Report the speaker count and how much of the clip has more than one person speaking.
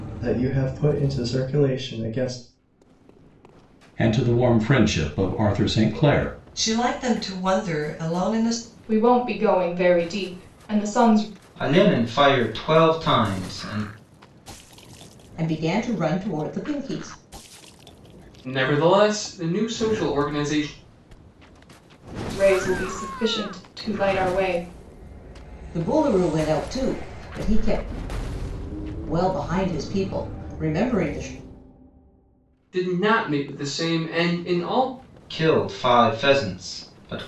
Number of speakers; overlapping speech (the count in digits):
7, no overlap